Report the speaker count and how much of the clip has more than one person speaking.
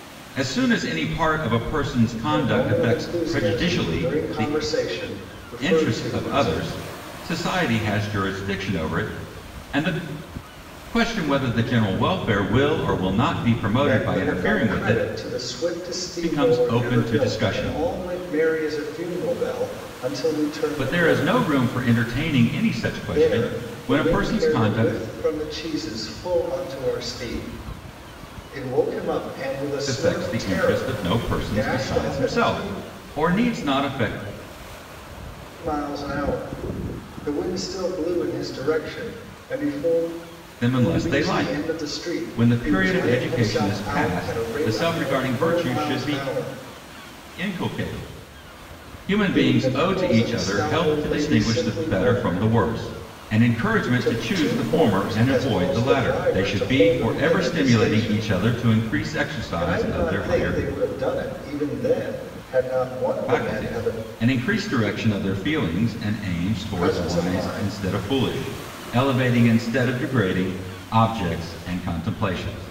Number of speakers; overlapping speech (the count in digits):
2, about 38%